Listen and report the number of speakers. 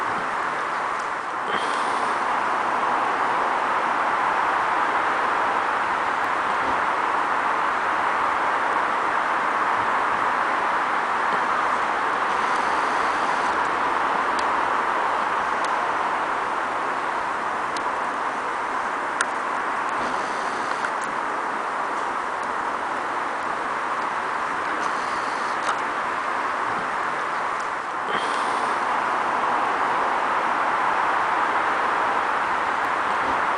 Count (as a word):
zero